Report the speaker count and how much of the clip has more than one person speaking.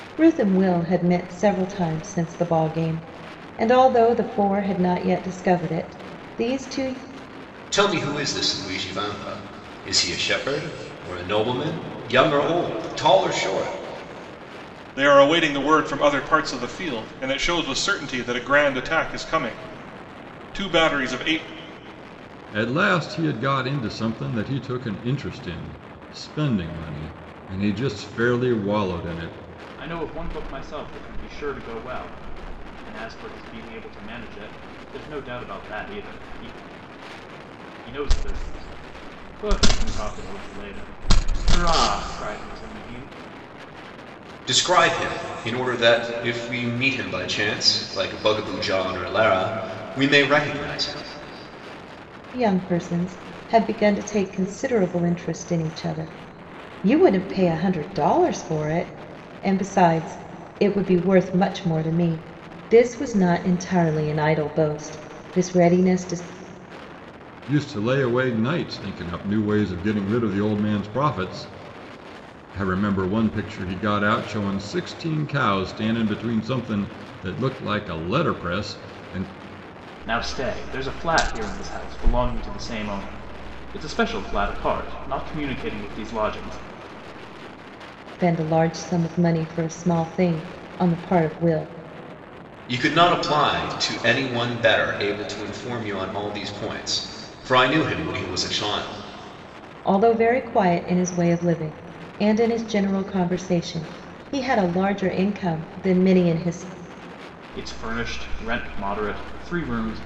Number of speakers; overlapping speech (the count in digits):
5, no overlap